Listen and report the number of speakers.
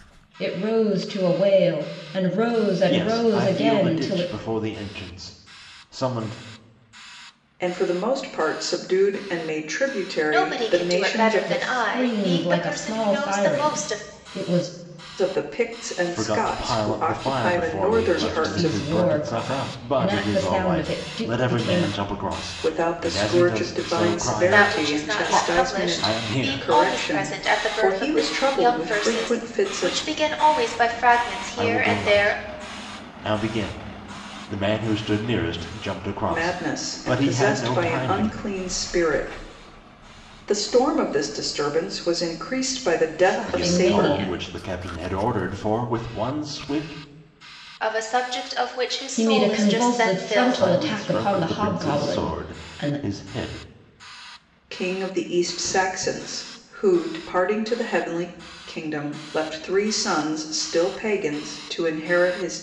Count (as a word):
four